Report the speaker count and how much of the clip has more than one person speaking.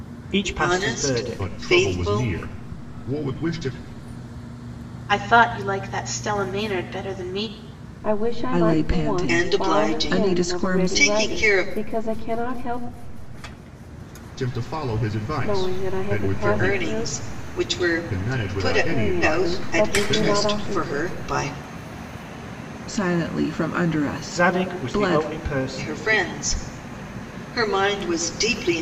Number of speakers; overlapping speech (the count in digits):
6, about 39%